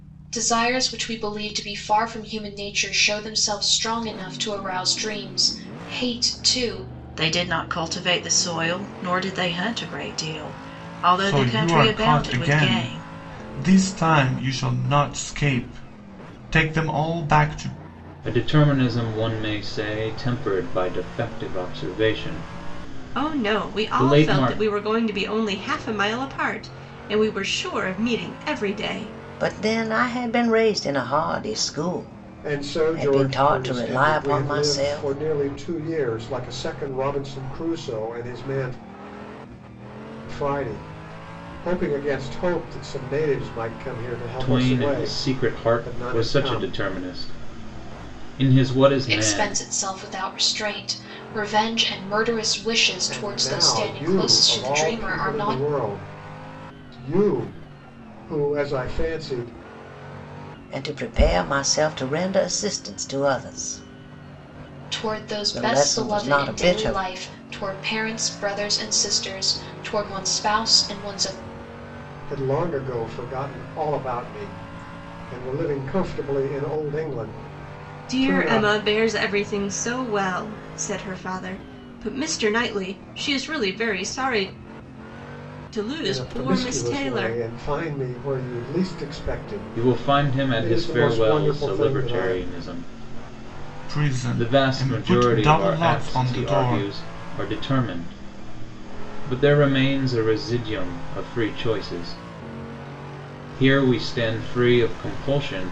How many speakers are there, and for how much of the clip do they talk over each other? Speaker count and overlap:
7, about 21%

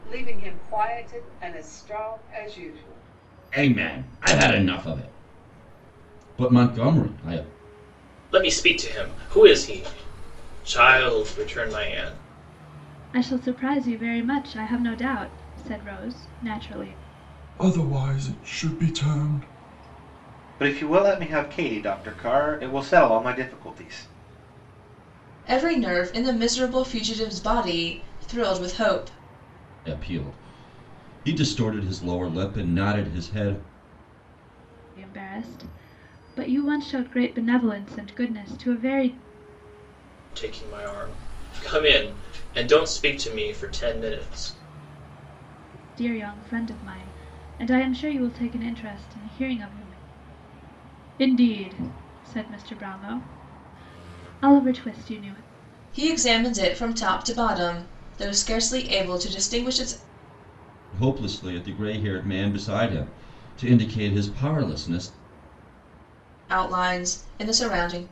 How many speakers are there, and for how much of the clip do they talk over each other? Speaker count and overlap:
7, no overlap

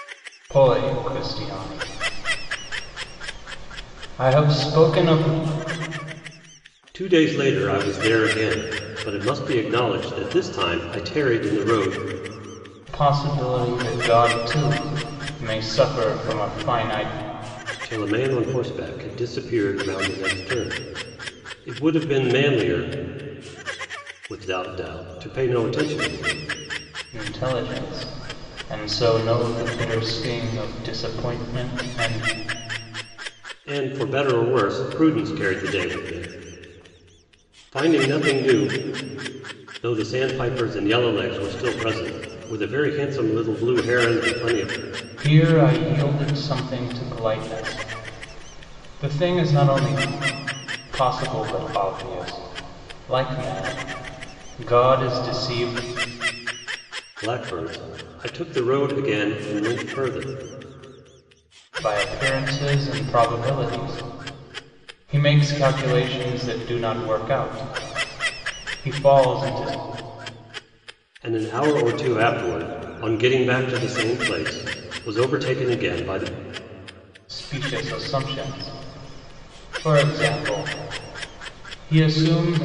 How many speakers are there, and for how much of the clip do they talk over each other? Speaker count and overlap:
2, no overlap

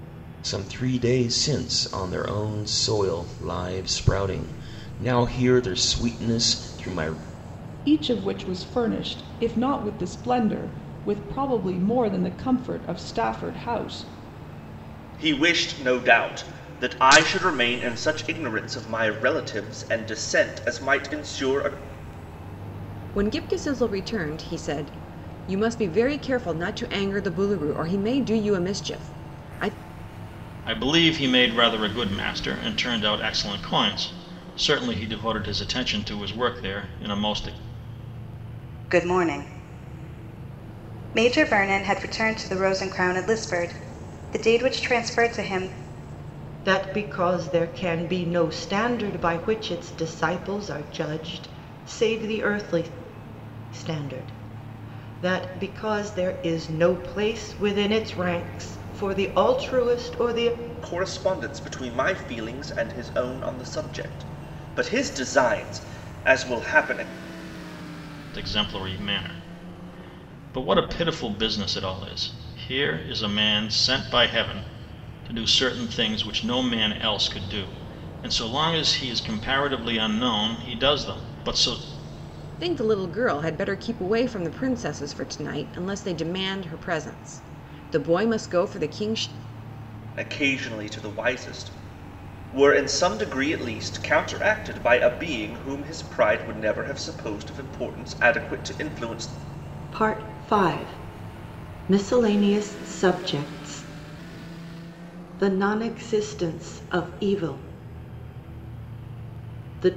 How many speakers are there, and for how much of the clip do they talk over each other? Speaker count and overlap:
7, no overlap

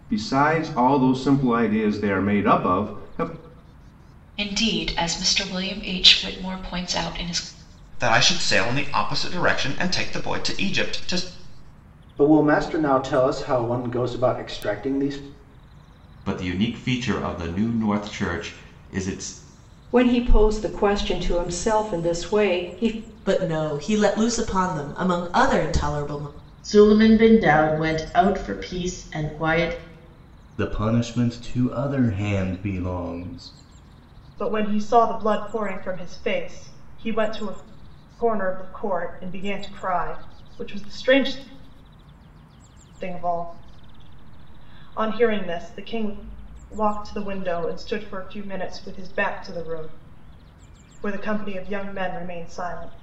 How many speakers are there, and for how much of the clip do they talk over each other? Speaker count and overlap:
10, no overlap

